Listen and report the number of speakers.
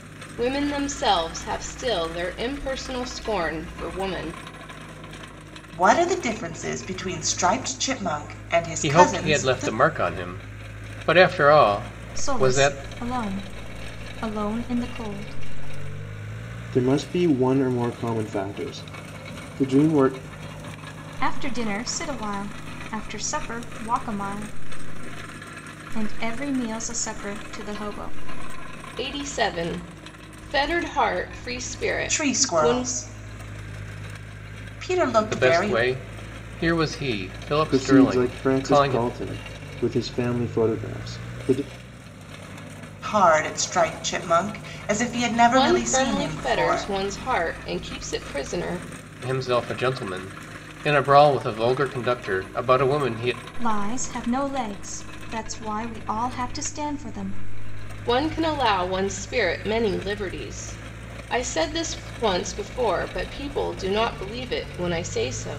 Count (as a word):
five